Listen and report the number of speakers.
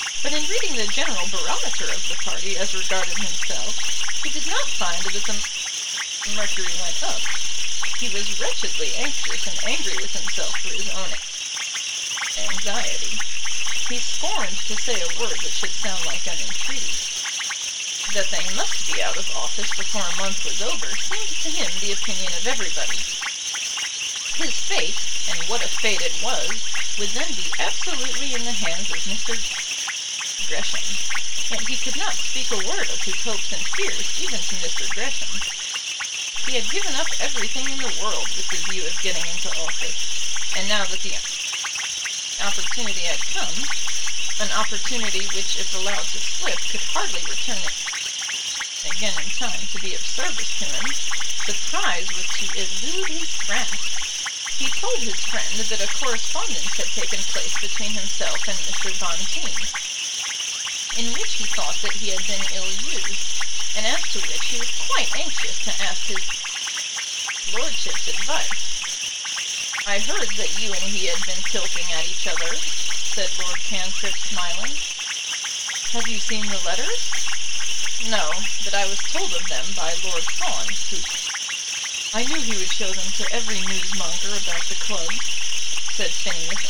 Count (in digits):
1